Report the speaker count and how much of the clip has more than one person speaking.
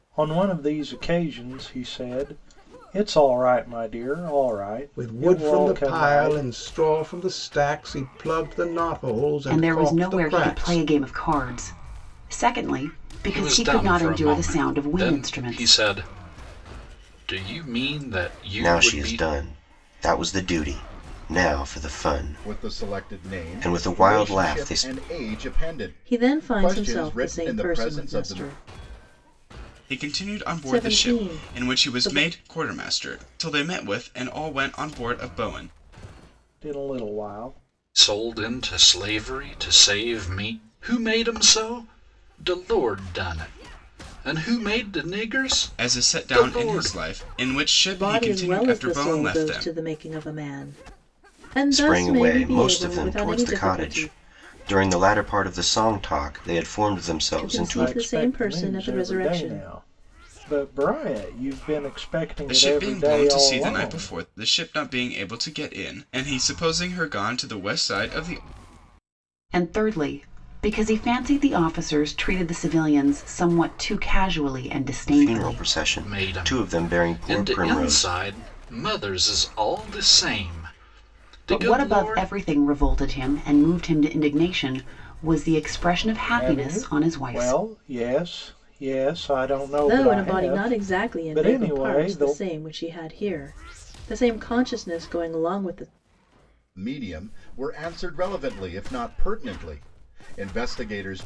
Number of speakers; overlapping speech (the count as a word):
eight, about 30%